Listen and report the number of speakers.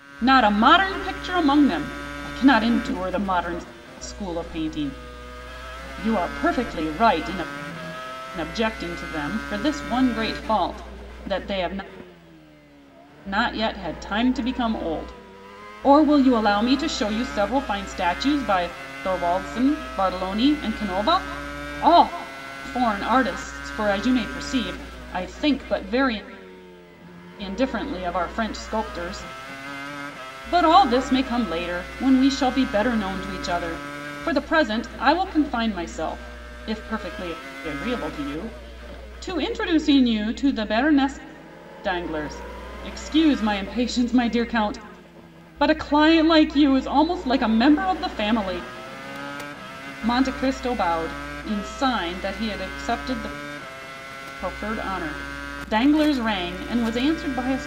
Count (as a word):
one